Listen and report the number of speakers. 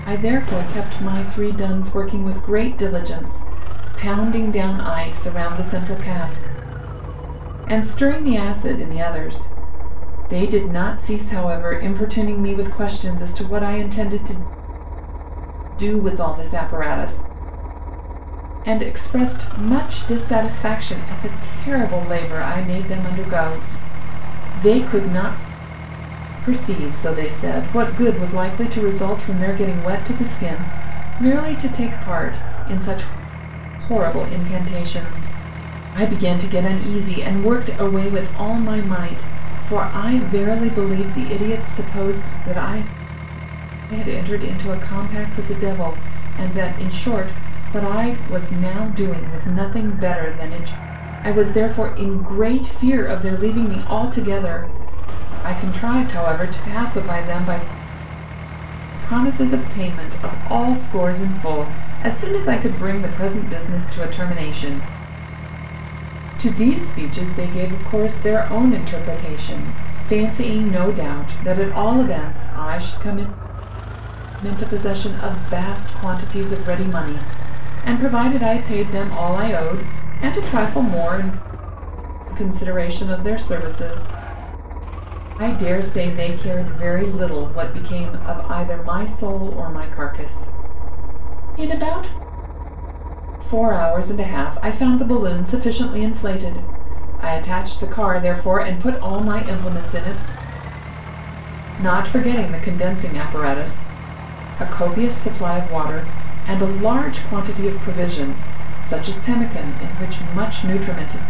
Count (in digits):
1